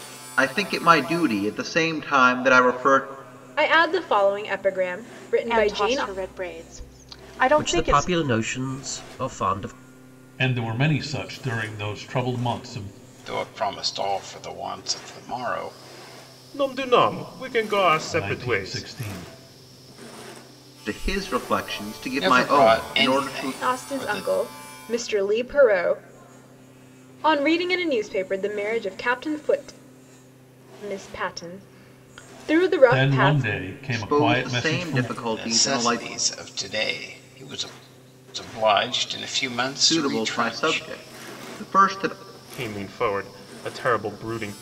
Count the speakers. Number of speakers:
7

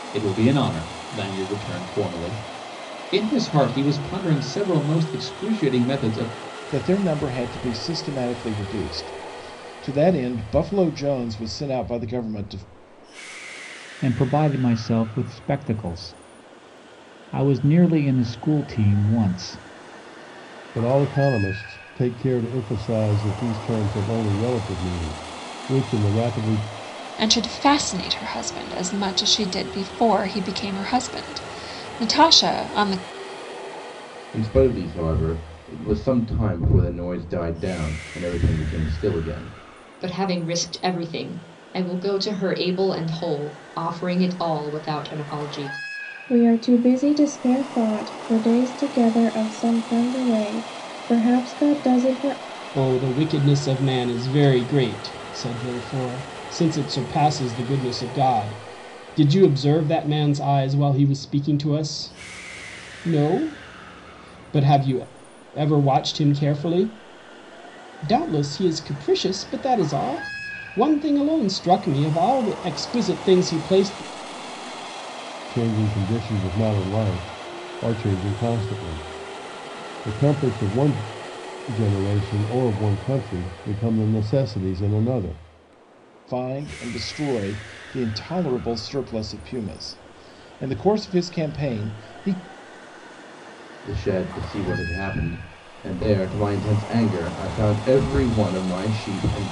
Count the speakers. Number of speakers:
9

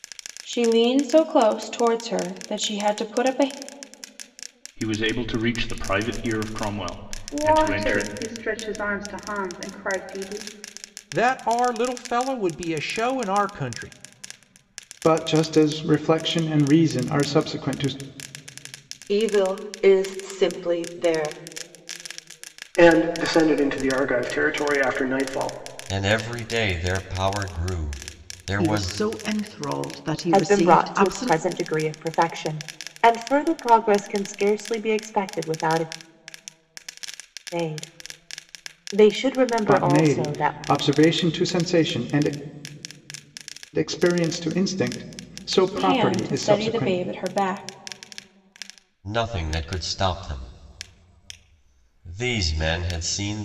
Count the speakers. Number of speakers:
10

